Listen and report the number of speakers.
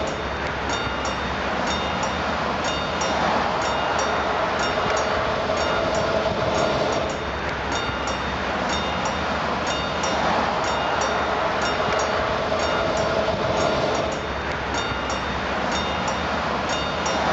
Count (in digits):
0